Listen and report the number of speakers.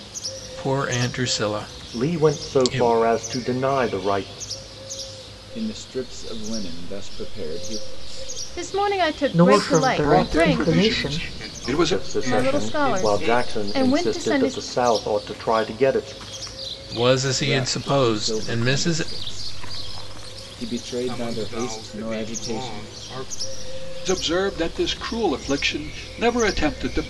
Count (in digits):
7